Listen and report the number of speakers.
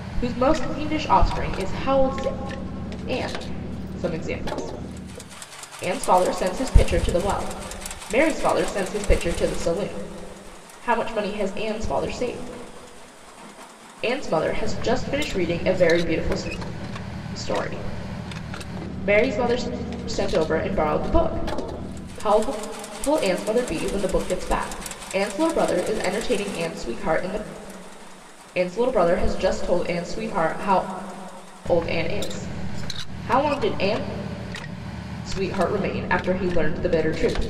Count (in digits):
1